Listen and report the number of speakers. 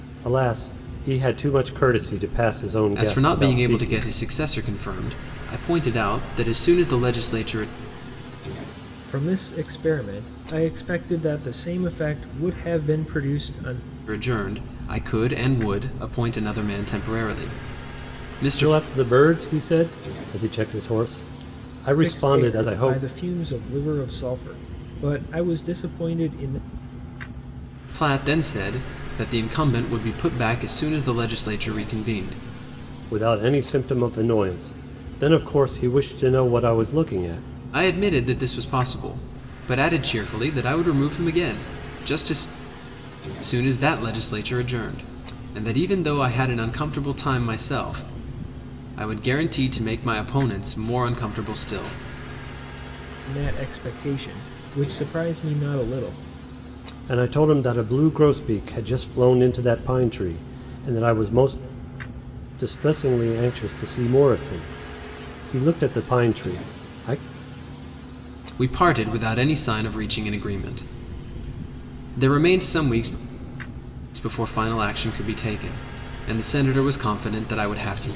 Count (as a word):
three